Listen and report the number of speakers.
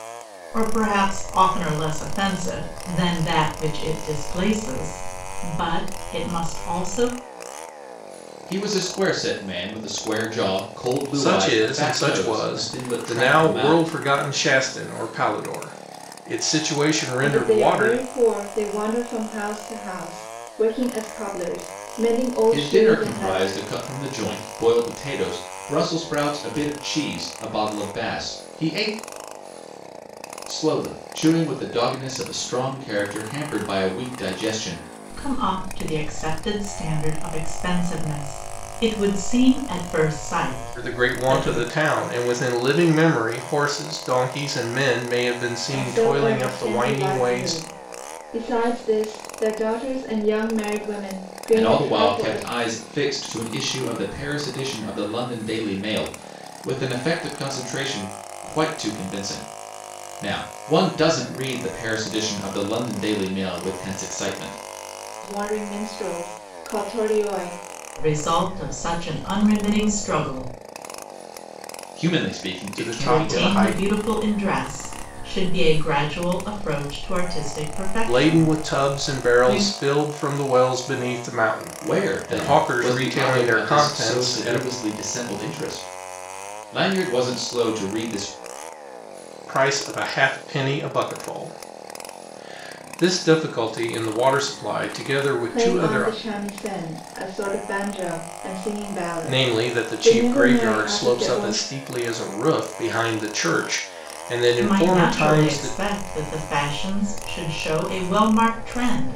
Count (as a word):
four